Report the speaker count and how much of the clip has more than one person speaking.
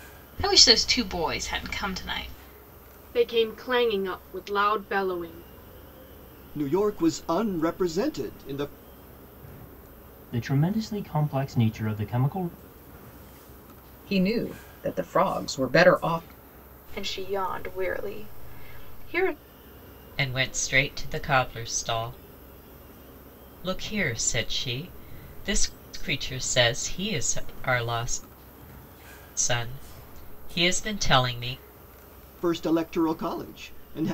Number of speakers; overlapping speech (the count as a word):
seven, no overlap